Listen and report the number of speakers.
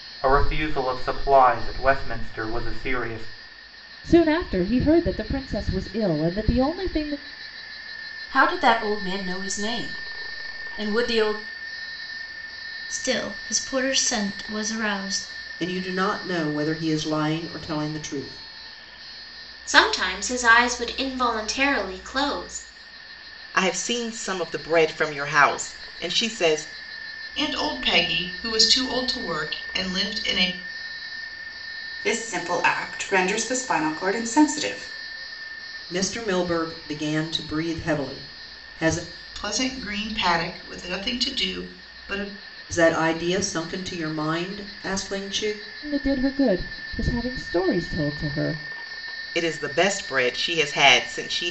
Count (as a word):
nine